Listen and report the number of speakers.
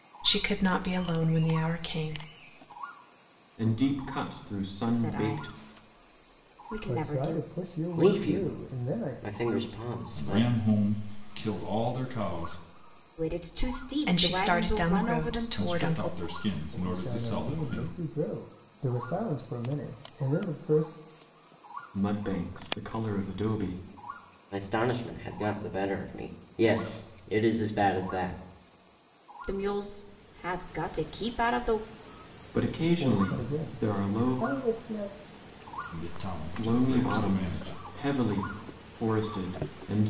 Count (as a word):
six